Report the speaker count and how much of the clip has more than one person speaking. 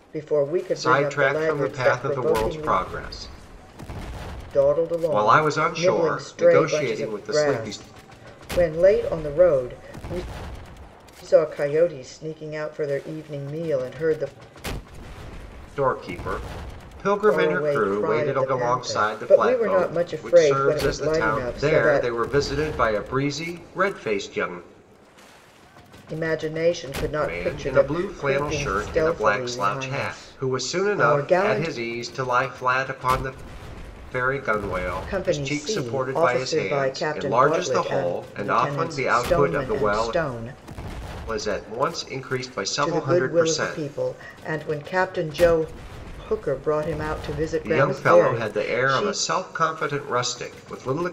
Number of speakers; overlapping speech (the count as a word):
two, about 43%